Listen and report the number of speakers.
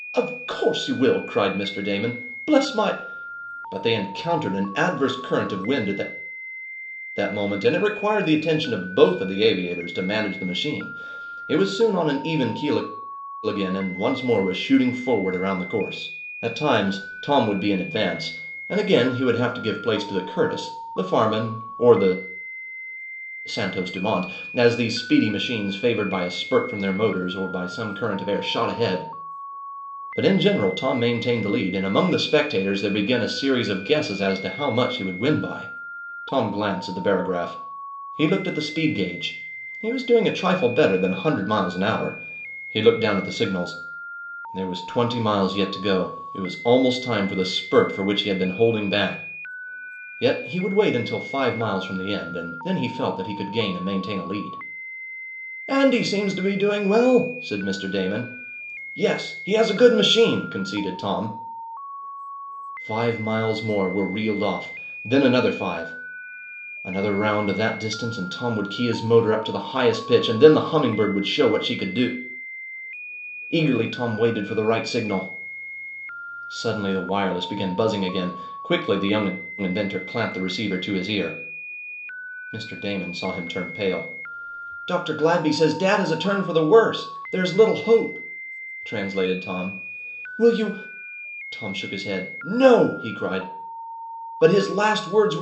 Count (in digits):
1